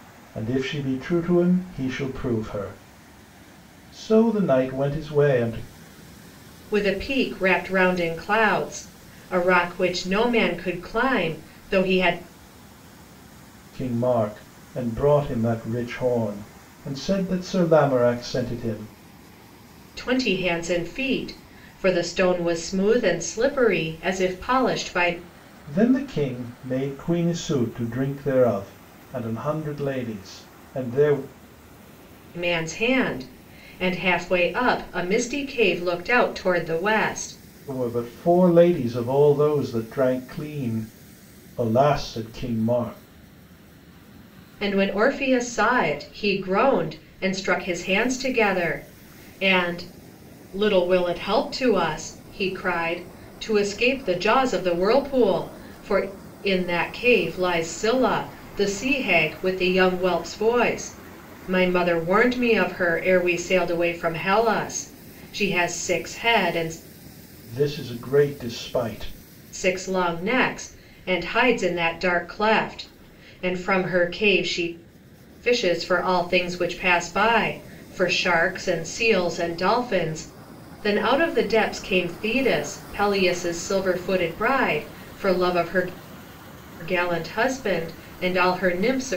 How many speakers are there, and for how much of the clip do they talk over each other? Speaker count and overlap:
2, no overlap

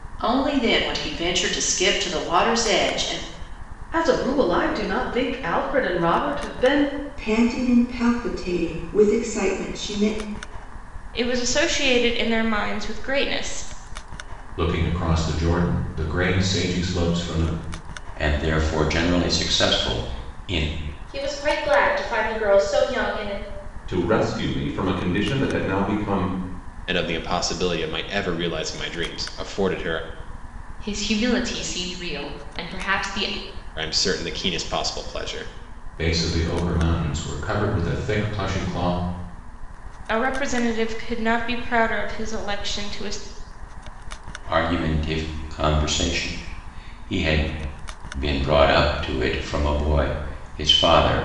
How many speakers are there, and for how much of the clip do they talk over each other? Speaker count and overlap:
10, no overlap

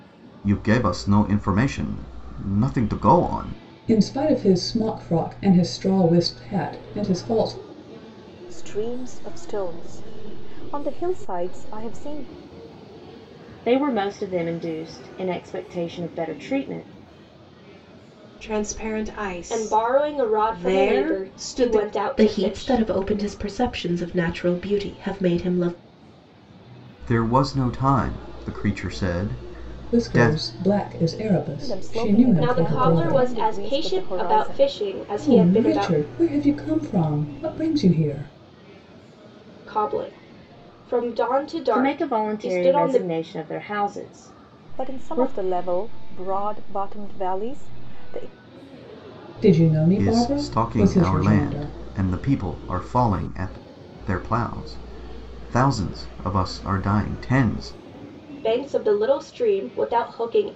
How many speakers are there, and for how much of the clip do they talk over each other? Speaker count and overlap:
7, about 19%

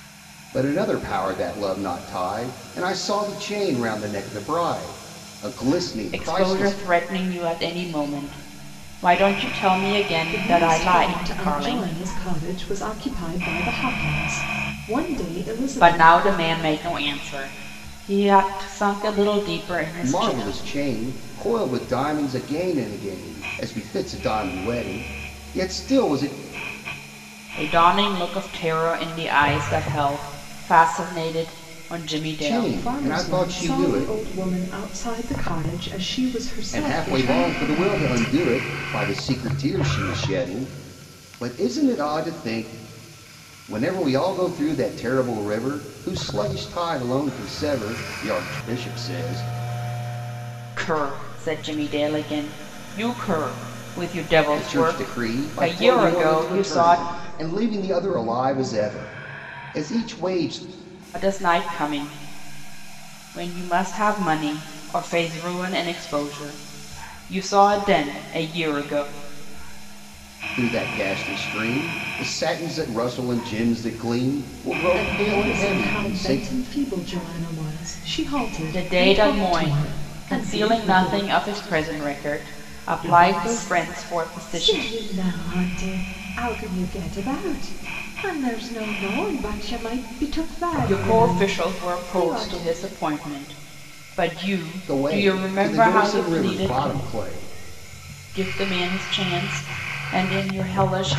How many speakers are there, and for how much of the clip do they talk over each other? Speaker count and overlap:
3, about 19%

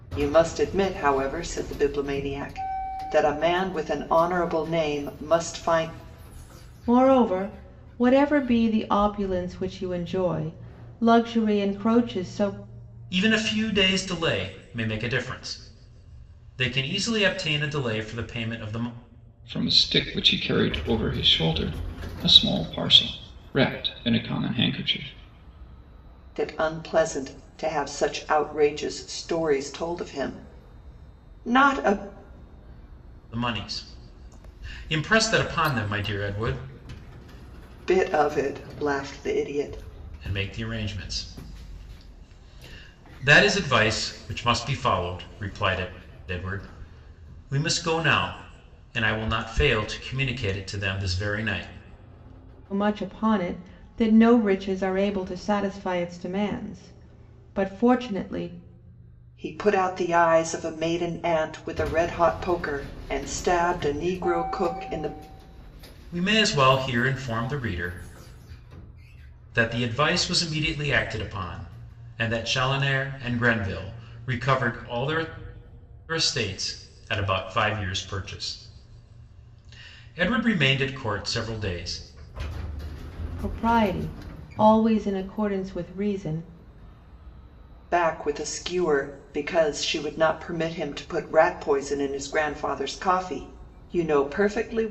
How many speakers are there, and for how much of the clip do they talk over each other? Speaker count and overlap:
4, no overlap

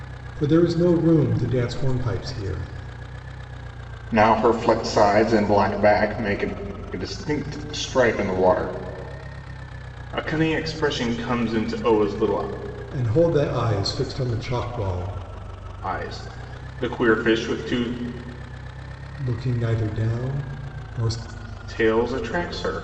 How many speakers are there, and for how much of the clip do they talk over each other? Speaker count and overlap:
2, no overlap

